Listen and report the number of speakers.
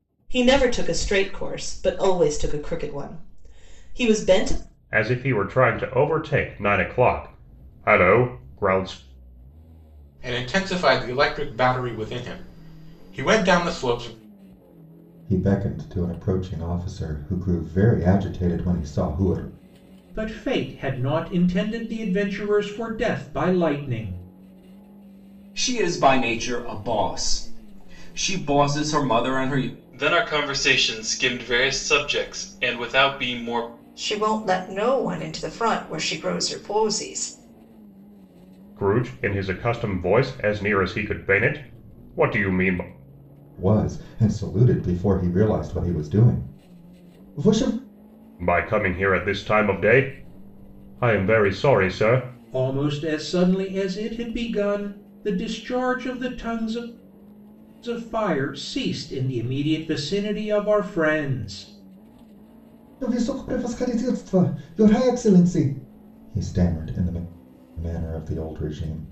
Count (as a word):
eight